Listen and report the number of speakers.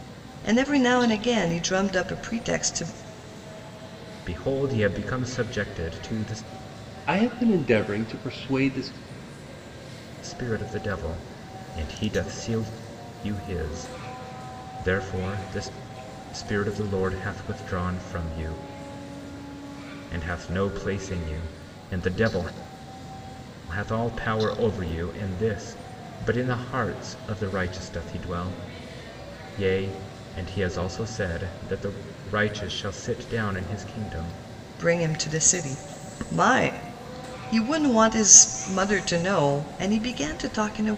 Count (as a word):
three